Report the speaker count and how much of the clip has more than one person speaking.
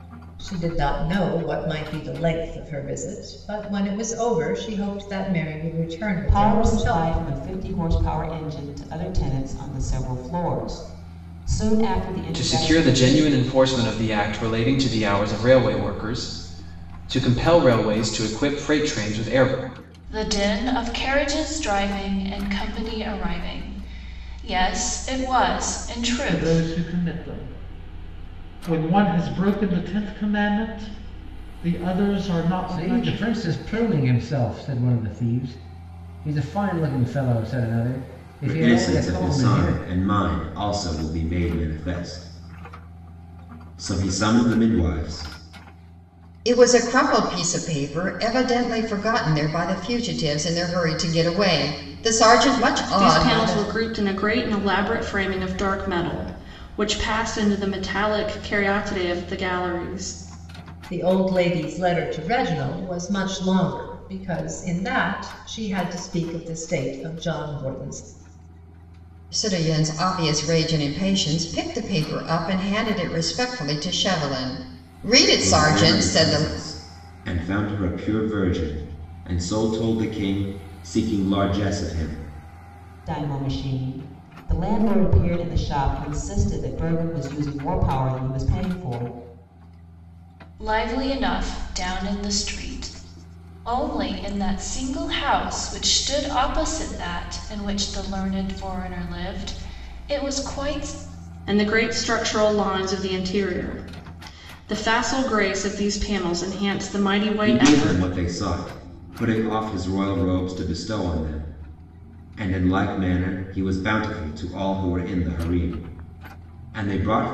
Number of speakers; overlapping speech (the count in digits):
9, about 6%